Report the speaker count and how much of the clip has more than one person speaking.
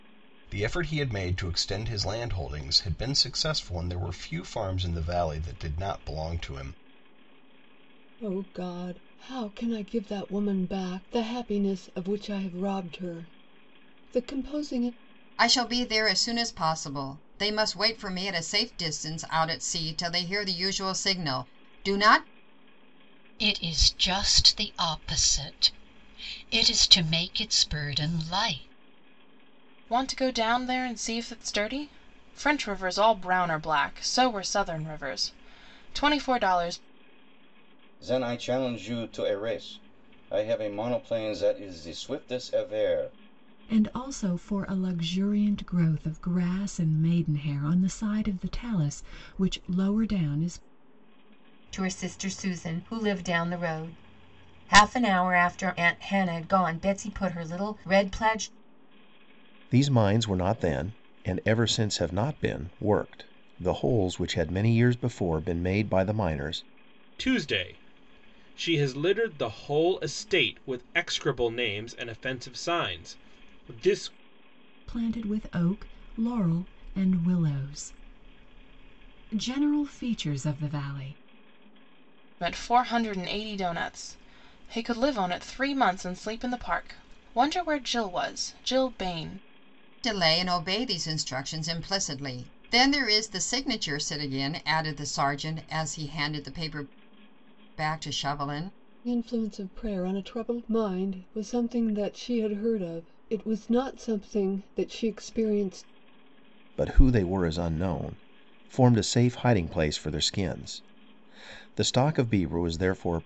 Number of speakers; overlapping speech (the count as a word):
ten, no overlap